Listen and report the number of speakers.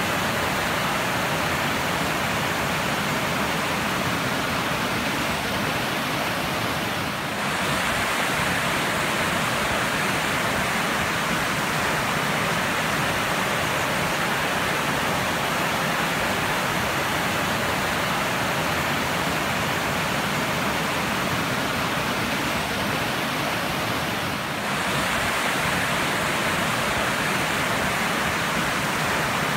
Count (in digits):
0